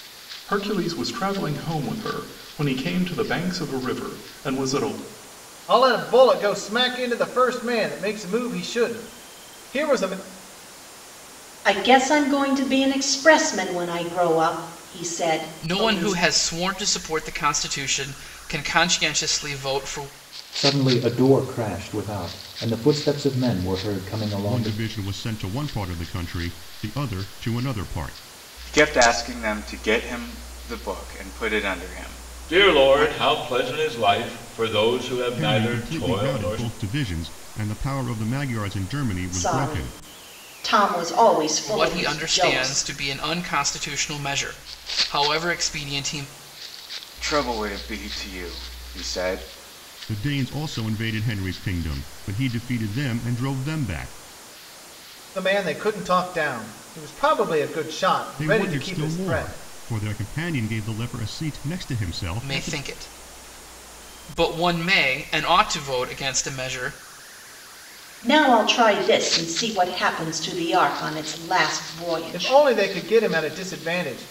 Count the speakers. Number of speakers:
8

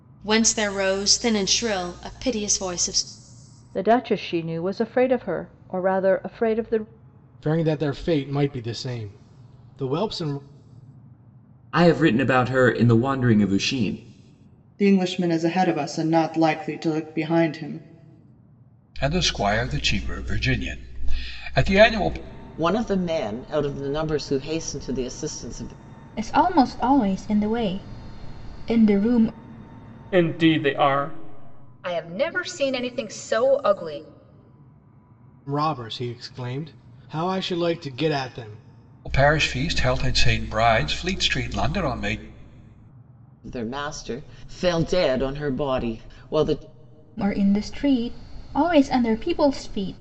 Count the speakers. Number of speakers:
10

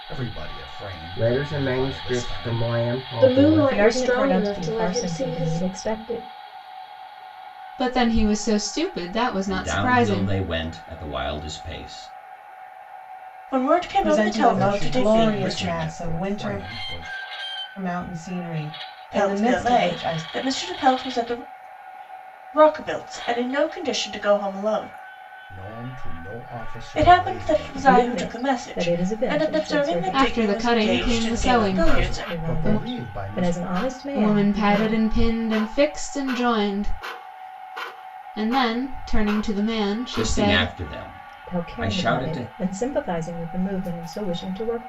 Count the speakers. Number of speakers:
8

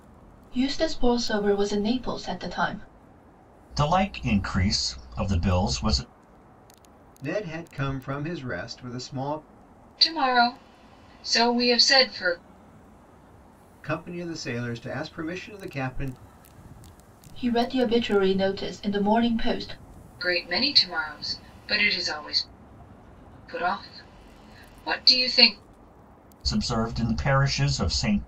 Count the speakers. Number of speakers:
4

